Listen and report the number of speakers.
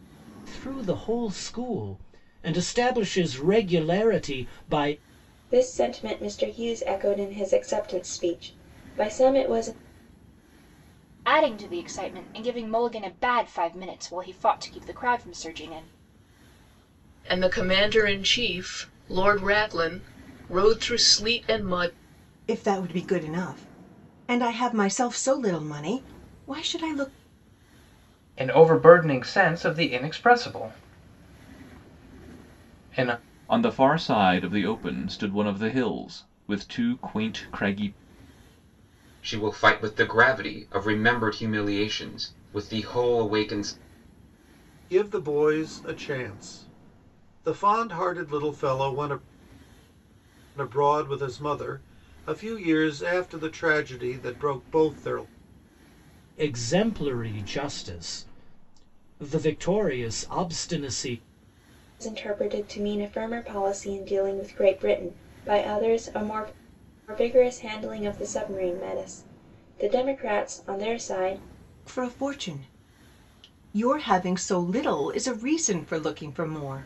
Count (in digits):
9